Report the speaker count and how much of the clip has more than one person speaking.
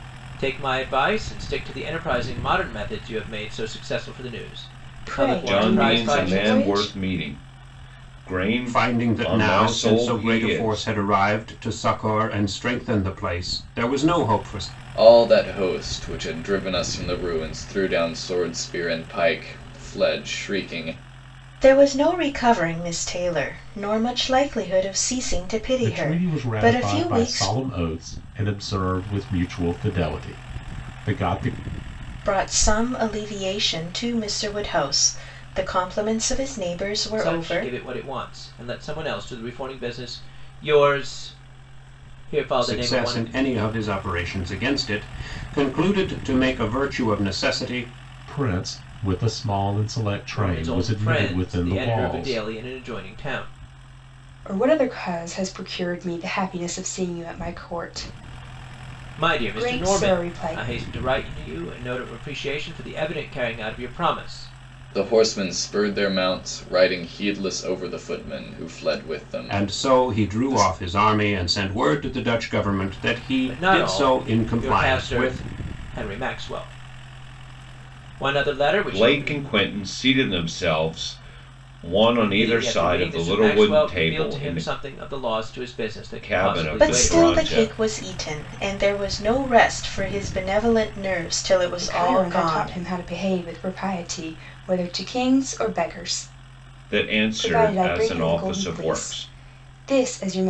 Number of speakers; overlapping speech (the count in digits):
7, about 22%